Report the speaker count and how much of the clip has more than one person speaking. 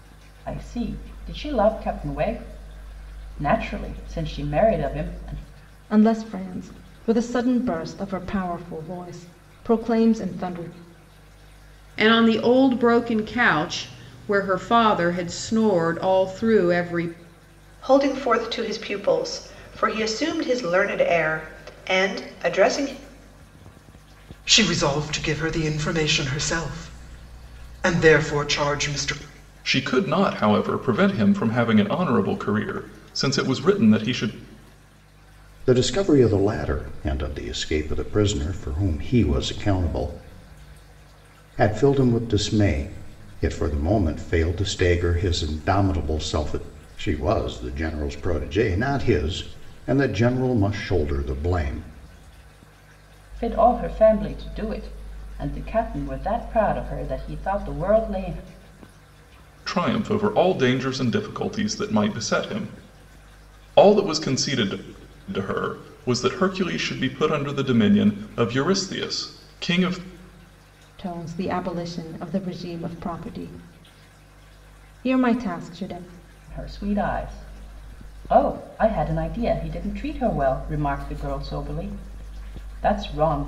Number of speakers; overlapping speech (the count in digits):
7, no overlap